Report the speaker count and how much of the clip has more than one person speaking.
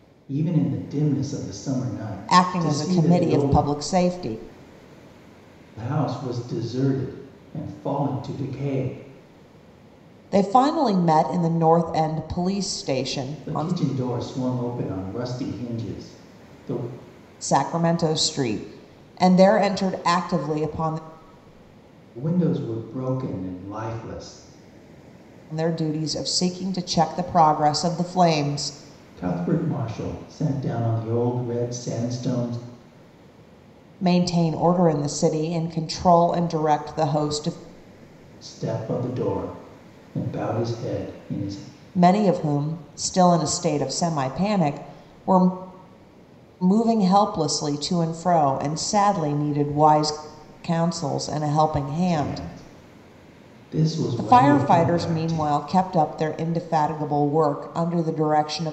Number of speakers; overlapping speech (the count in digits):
2, about 6%